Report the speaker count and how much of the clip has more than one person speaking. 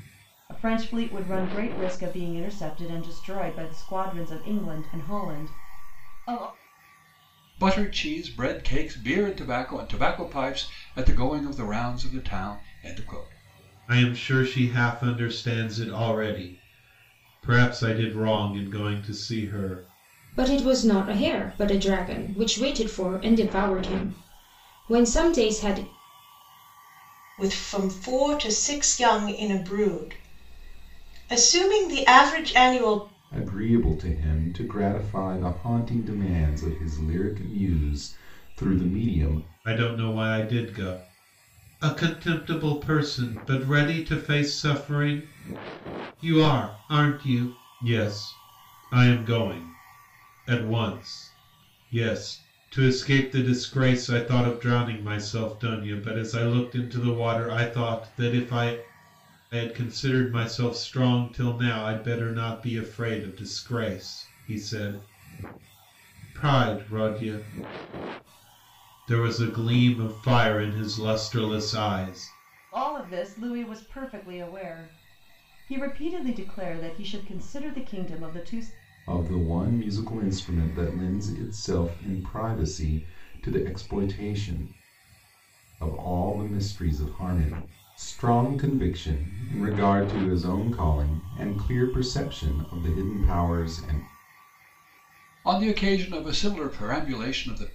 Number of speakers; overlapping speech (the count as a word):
six, no overlap